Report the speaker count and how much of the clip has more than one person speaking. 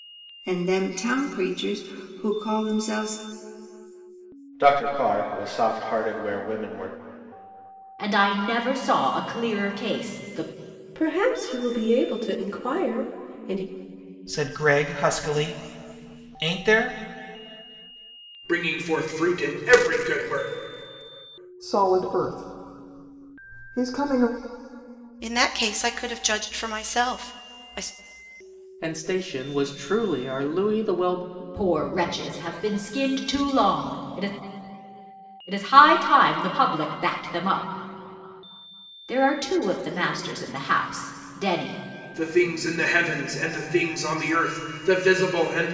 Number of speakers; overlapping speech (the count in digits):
9, no overlap